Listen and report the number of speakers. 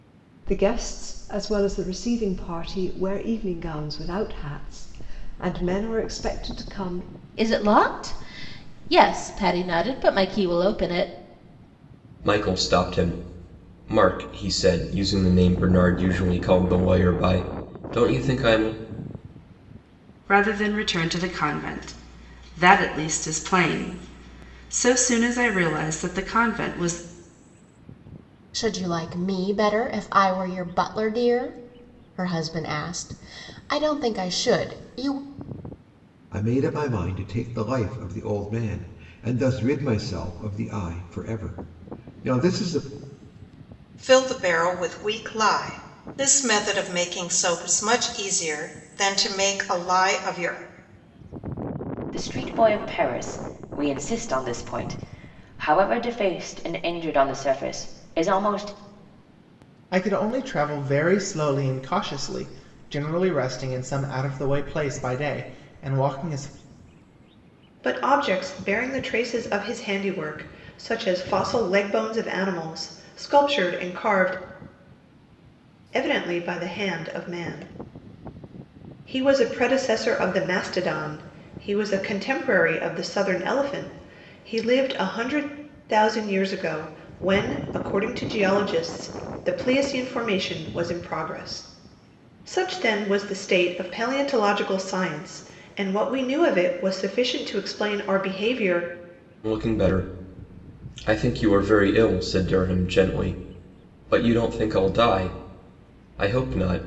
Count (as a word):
ten